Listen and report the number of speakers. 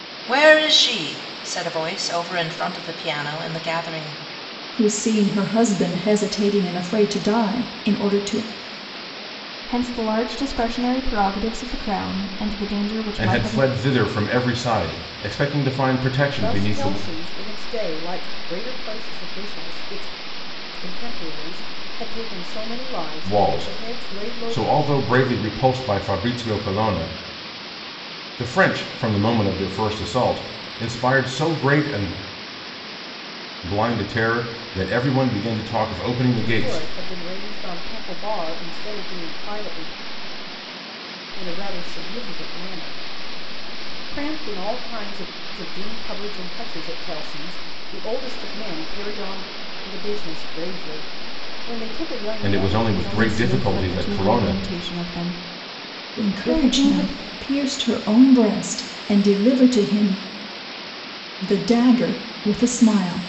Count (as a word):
five